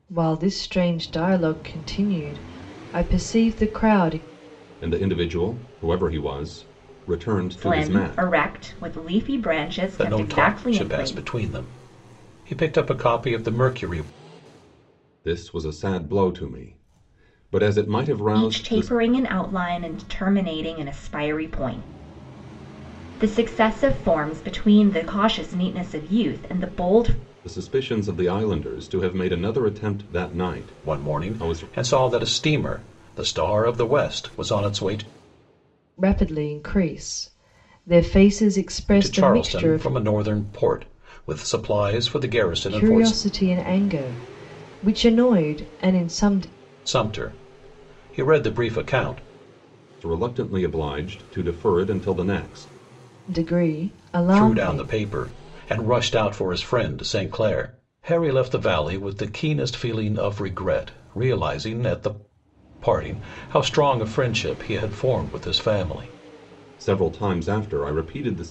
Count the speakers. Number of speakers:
four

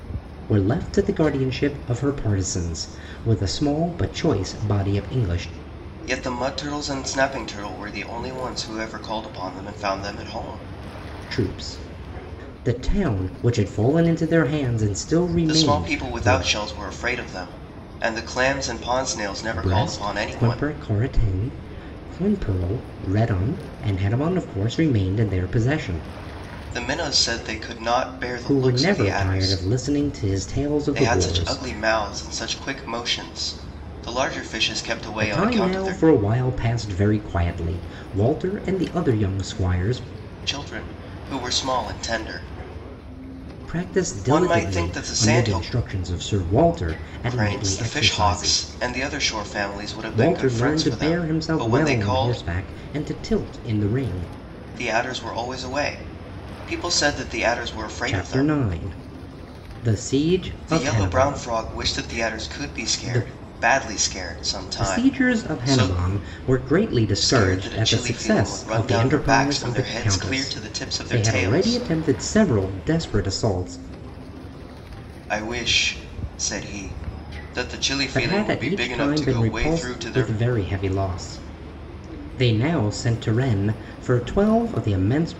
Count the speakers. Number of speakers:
two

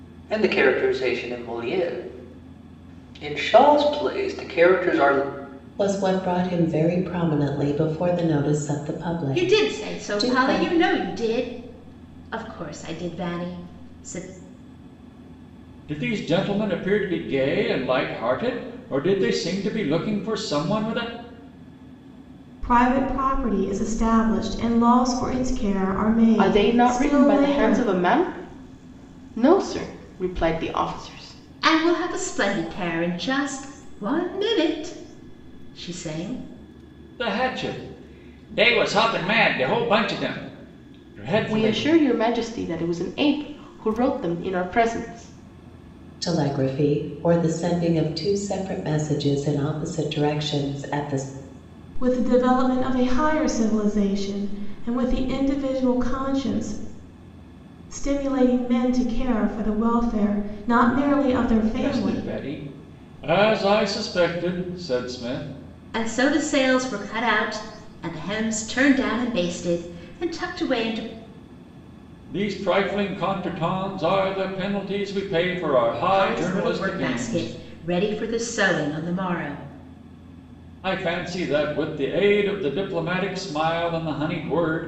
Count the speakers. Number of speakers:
six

